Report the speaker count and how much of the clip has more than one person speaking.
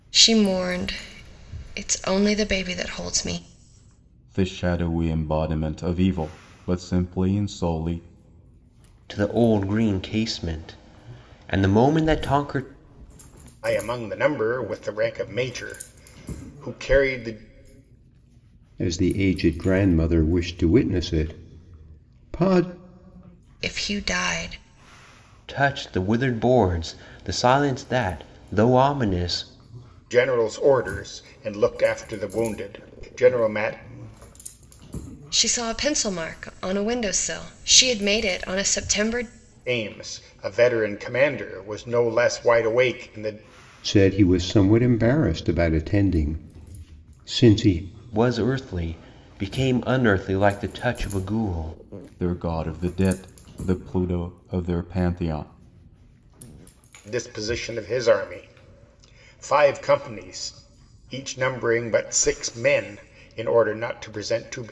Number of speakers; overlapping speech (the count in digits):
5, no overlap